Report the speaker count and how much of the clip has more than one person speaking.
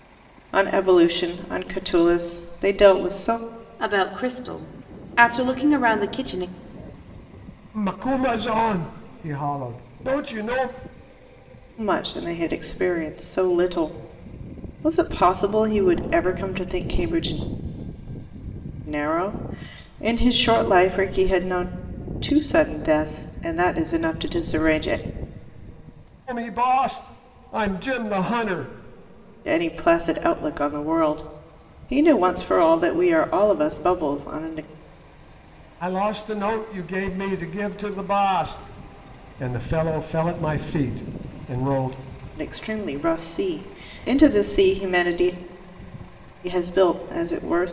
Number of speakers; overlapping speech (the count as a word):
three, no overlap